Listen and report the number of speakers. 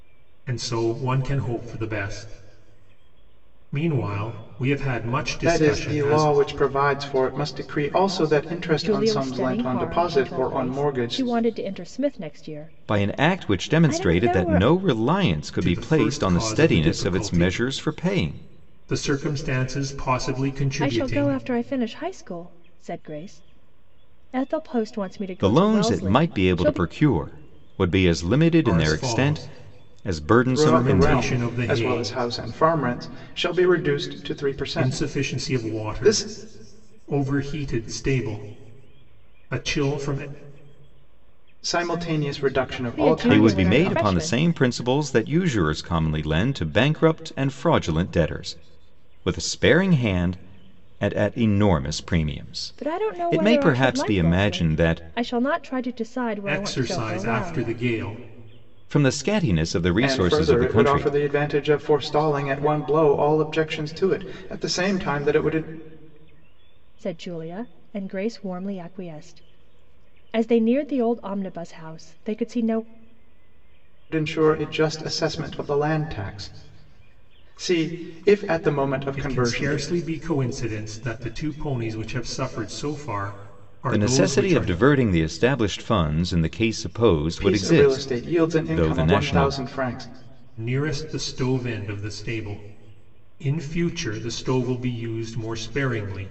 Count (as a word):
four